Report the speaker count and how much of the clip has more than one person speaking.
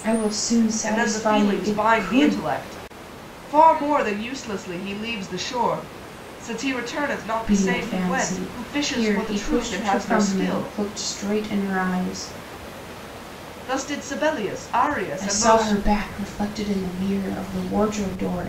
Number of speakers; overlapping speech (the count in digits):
2, about 30%